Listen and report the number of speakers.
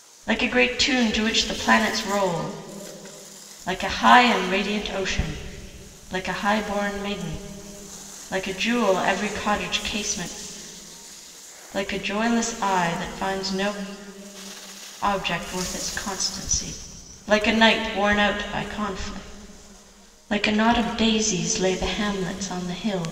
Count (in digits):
1